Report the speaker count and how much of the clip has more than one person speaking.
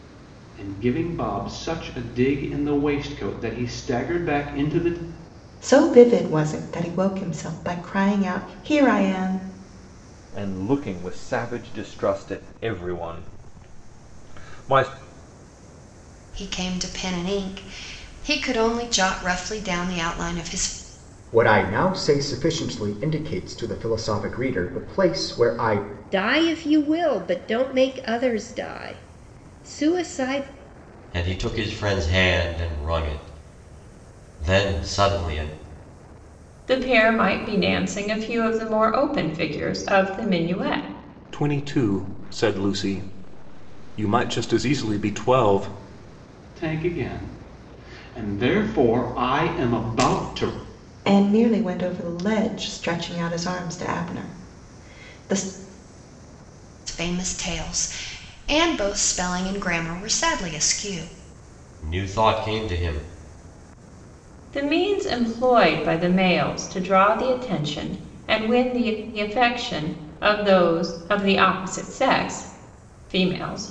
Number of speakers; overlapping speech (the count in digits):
9, no overlap